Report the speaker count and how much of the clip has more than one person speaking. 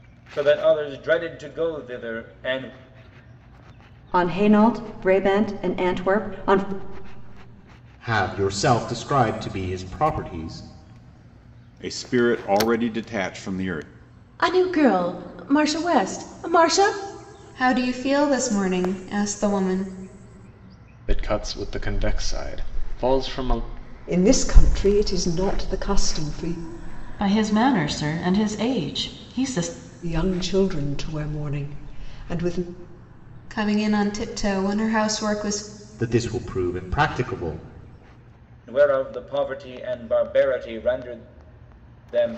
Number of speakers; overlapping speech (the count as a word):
nine, no overlap